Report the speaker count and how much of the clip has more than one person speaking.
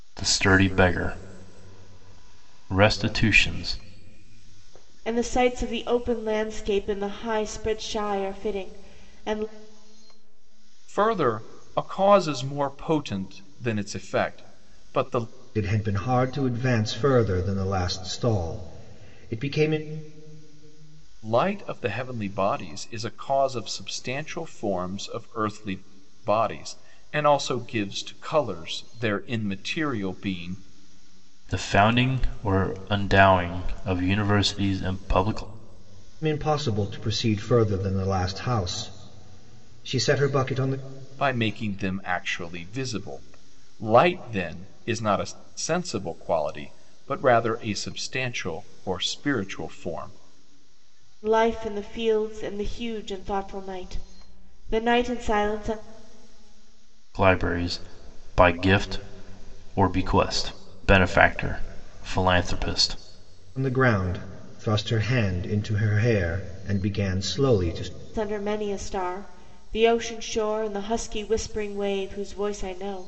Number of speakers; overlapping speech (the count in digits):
4, no overlap